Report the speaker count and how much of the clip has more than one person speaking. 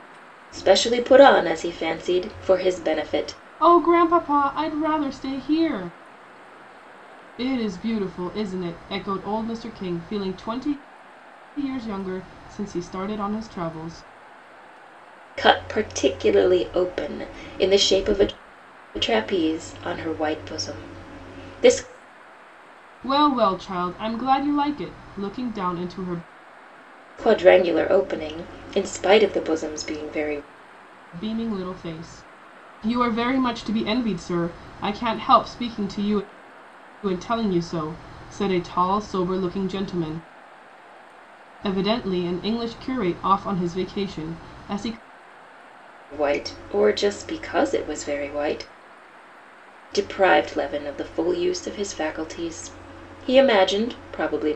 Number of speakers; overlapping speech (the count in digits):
2, no overlap